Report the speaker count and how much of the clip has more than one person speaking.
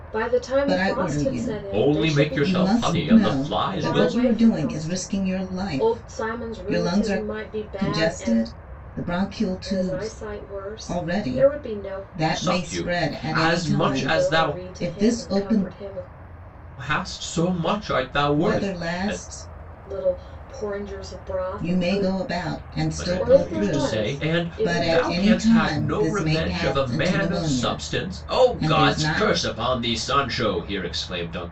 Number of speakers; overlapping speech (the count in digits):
3, about 65%